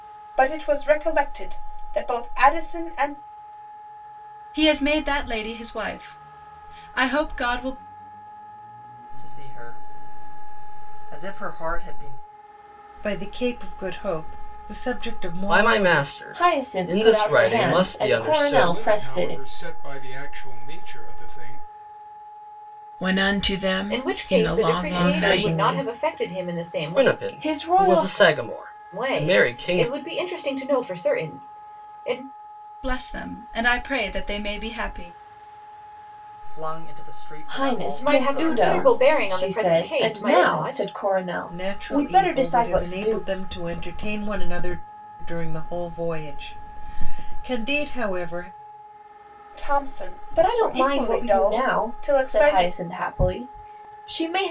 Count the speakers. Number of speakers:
9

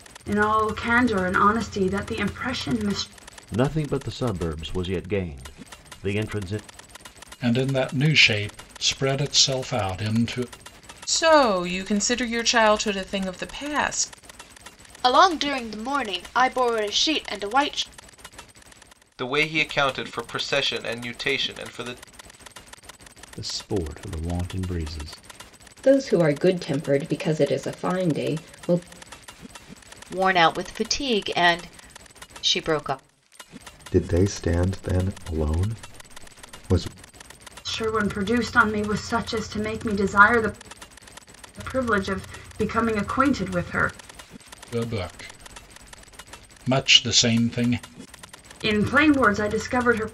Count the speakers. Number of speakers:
10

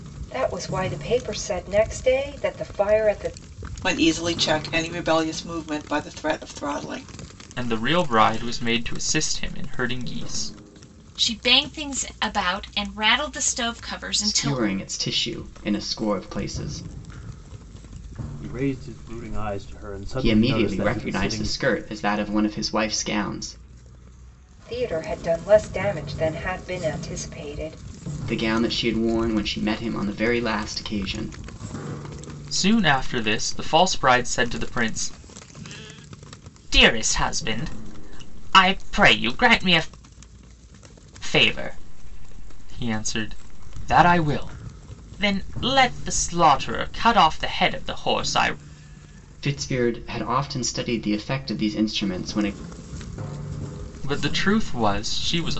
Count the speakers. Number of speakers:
6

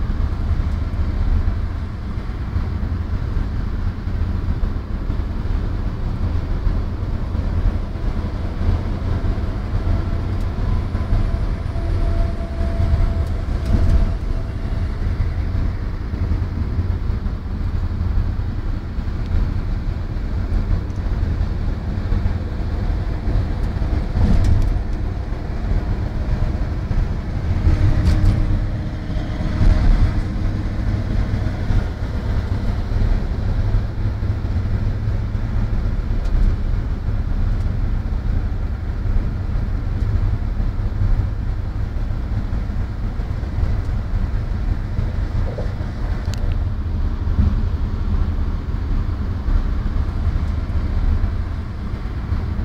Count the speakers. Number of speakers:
0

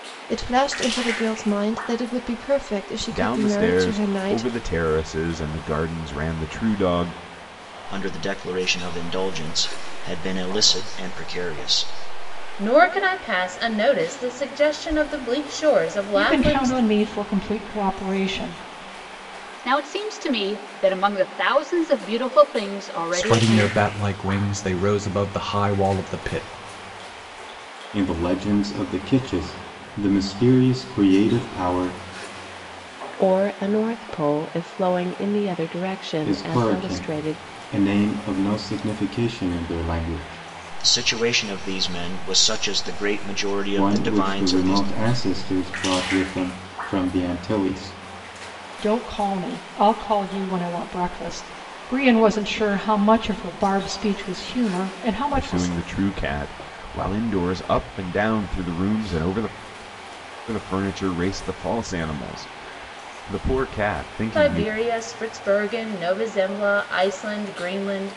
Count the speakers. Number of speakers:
9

